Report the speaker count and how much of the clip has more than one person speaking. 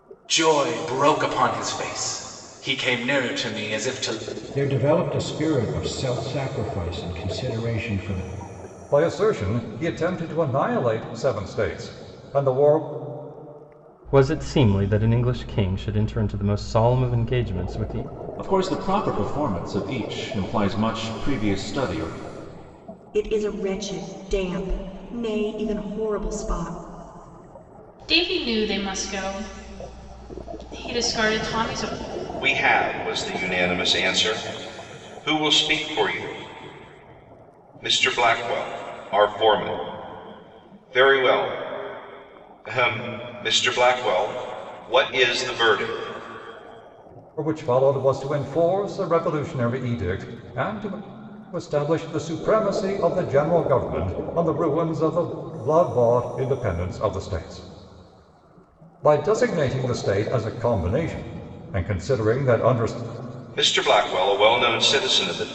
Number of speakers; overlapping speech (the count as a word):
eight, no overlap